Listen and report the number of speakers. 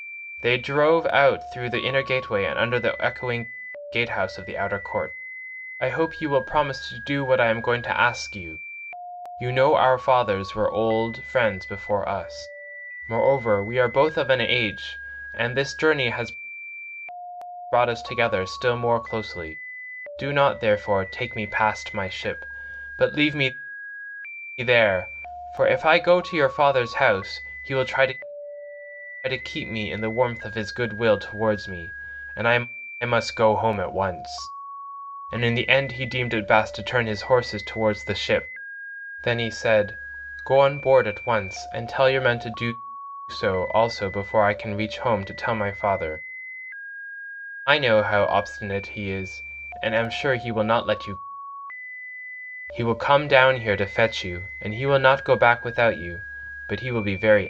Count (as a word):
one